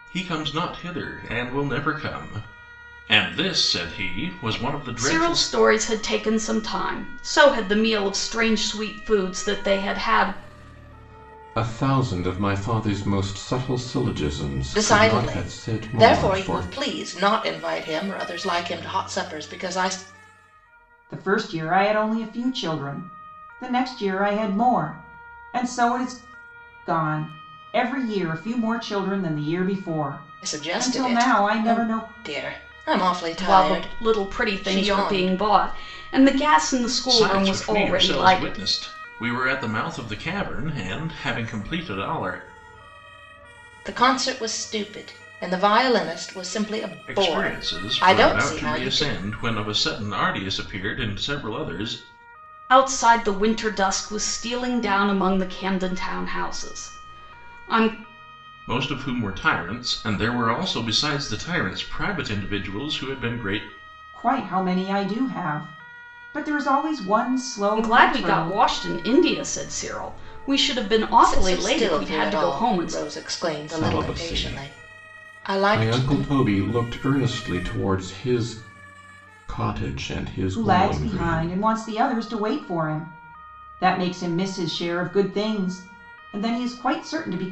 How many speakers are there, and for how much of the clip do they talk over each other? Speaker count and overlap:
5, about 18%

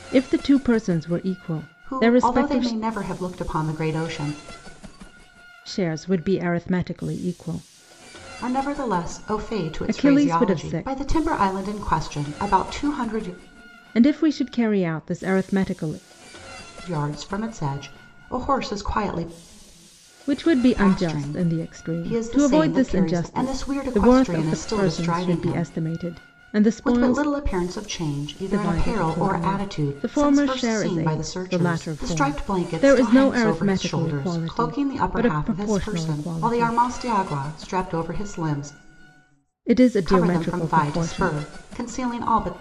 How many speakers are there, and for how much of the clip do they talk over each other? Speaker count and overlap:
2, about 39%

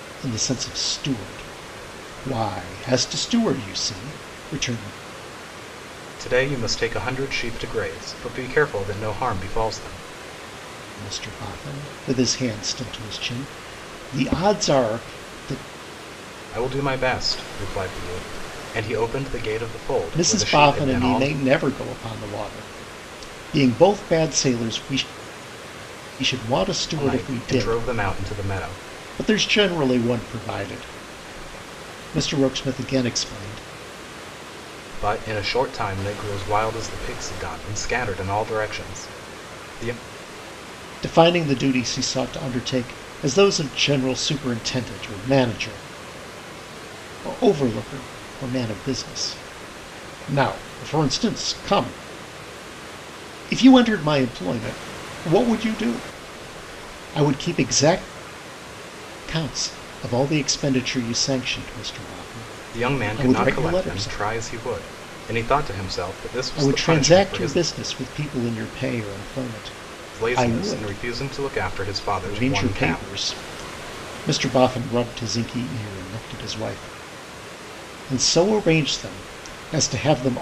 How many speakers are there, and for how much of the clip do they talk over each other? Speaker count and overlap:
2, about 8%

